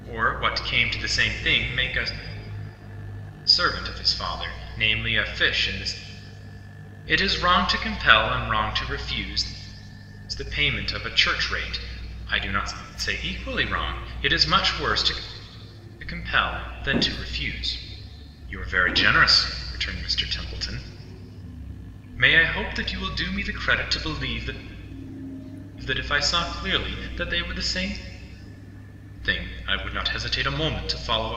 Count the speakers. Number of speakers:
1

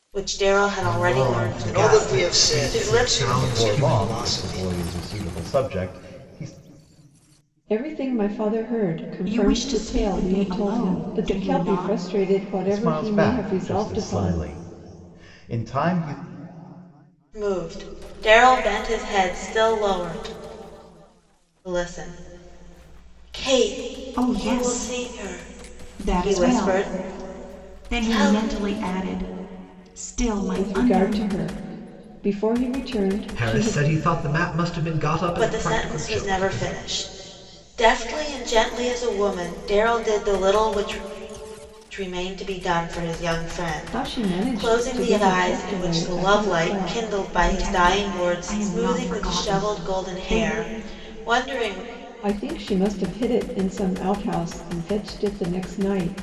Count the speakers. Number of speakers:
6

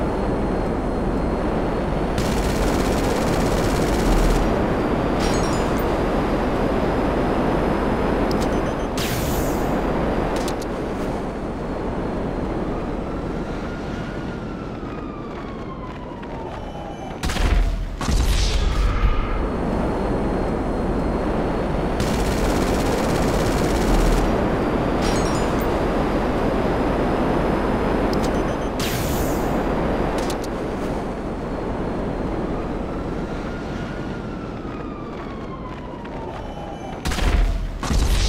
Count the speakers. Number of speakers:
0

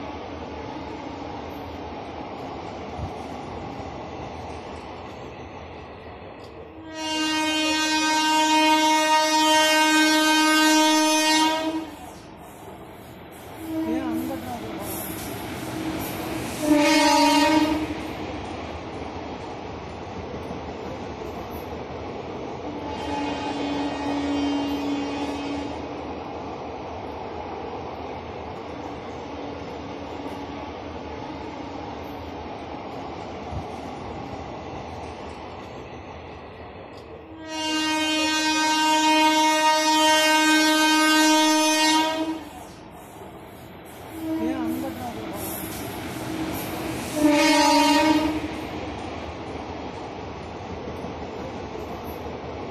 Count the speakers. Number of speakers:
0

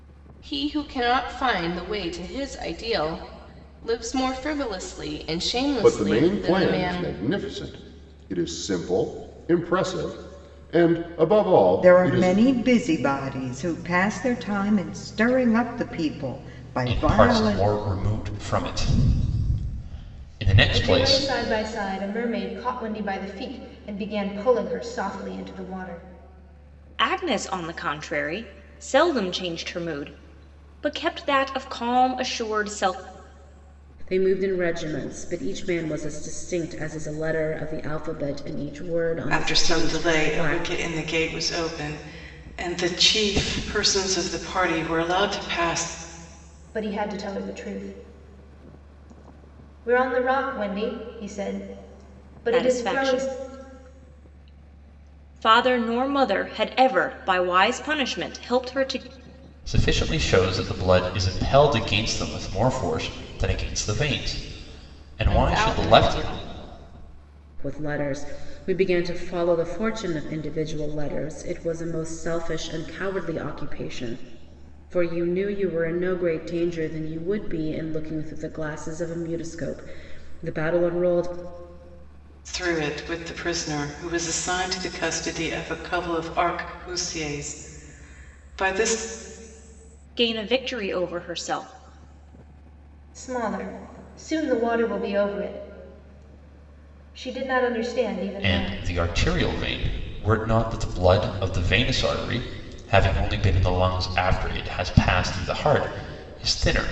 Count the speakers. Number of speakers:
8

